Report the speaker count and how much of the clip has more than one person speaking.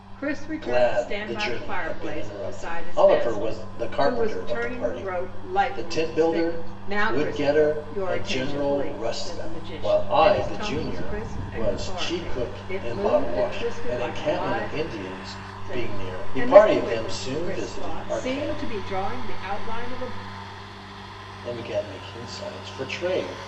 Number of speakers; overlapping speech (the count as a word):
two, about 70%